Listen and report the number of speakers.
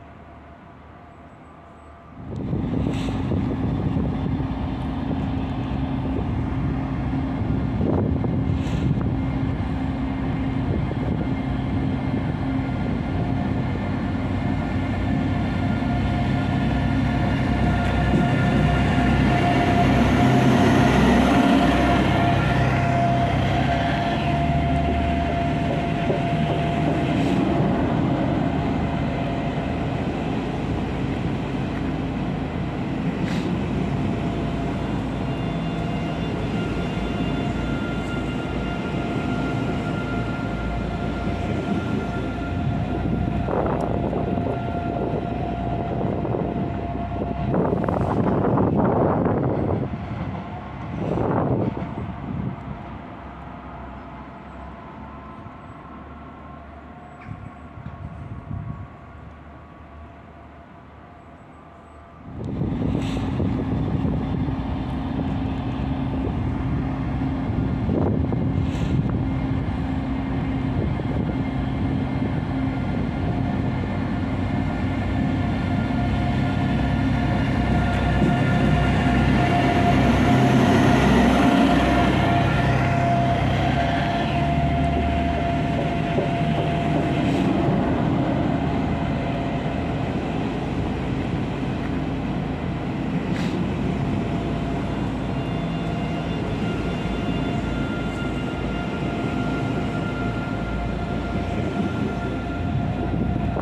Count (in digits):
0